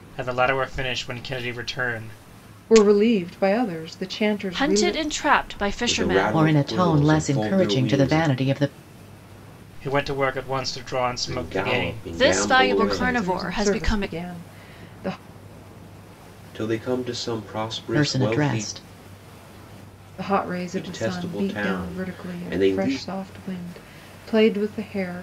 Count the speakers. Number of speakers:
5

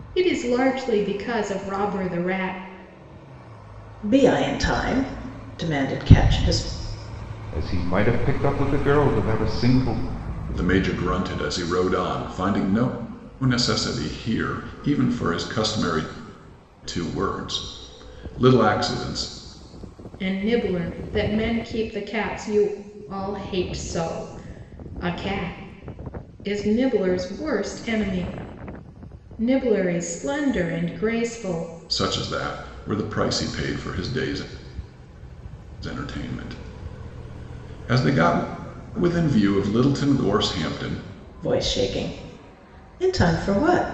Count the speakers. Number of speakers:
4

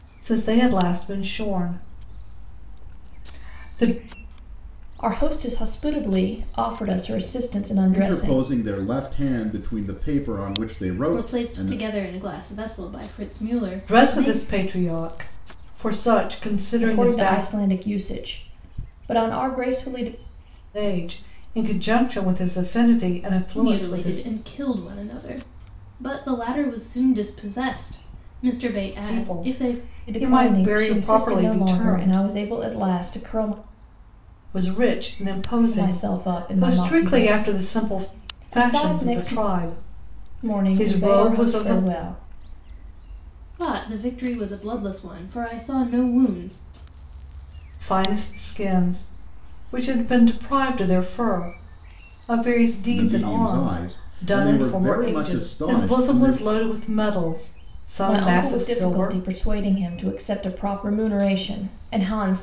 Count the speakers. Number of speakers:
4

